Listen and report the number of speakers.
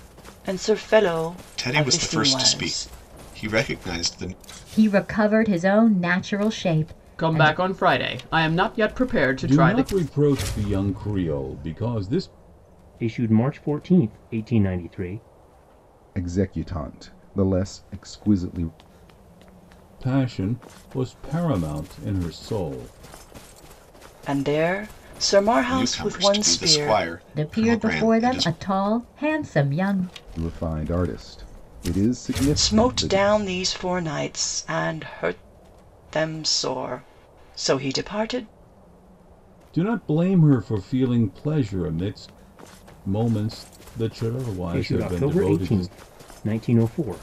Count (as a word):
seven